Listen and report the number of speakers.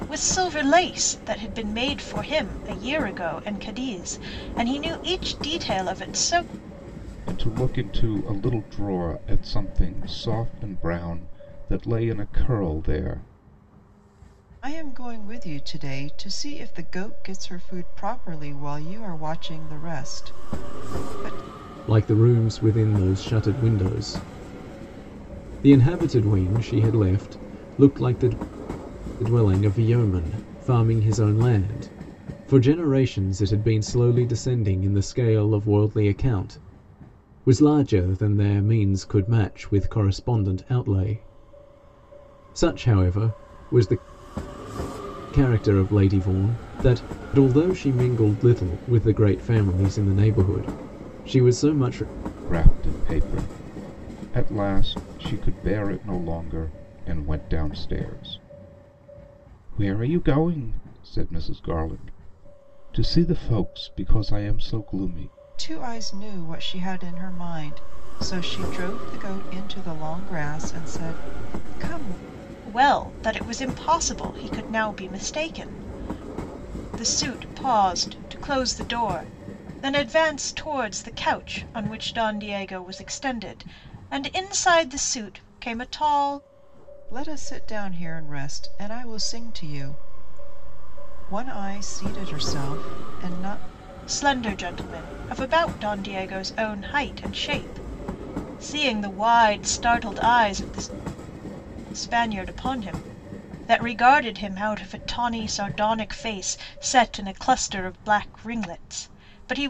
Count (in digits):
4